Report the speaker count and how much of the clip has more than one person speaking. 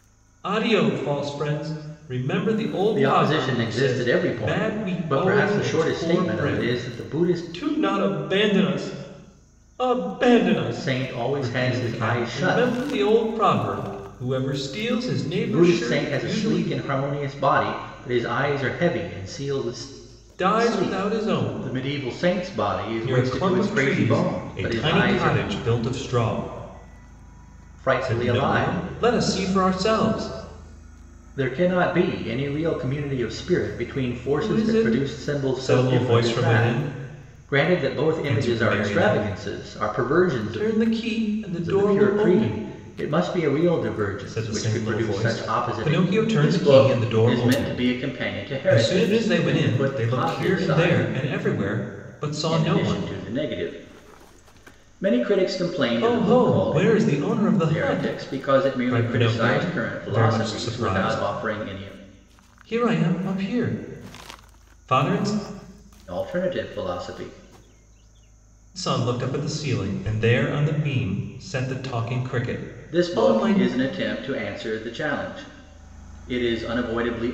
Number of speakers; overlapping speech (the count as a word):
two, about 41%